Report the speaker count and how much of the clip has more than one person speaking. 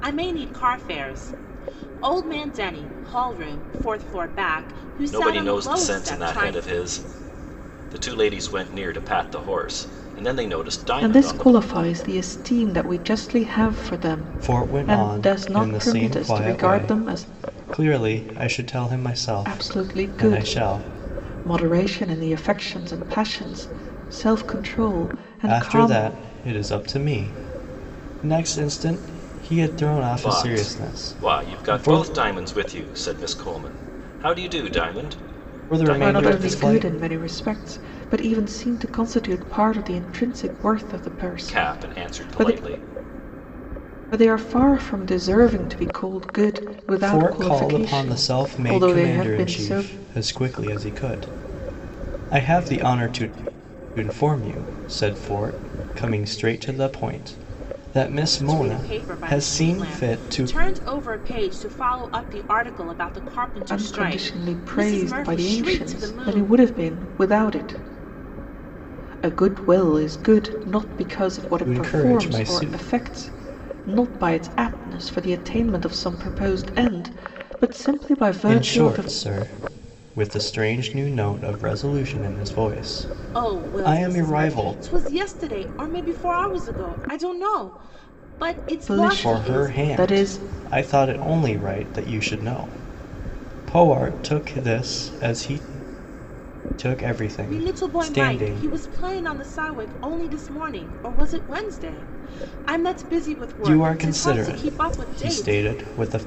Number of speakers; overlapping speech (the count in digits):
4, about 26%